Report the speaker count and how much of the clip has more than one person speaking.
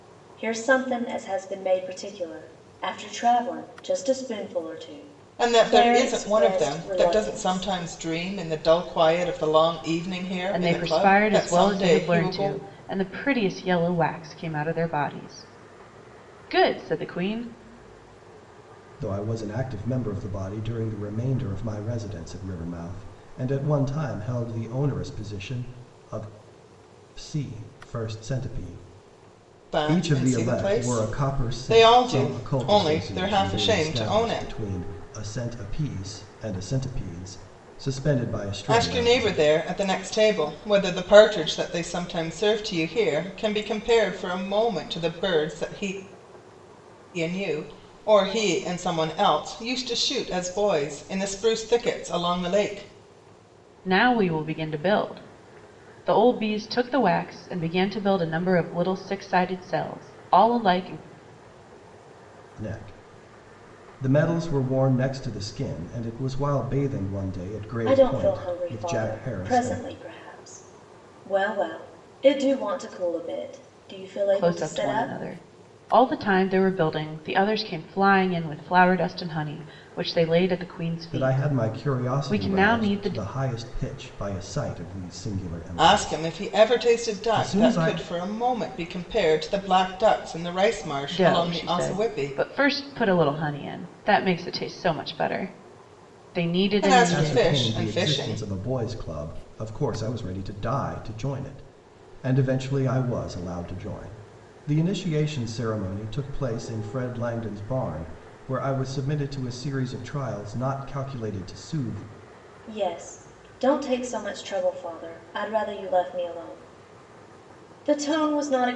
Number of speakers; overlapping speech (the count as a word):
four, about 17%